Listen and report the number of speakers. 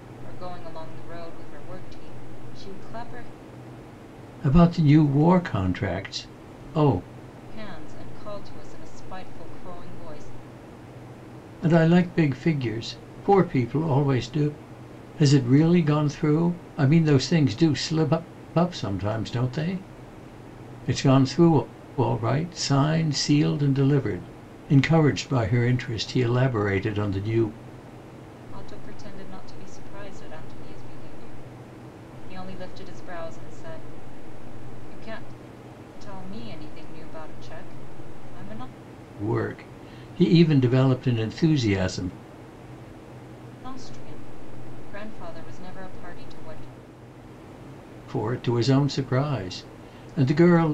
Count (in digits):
2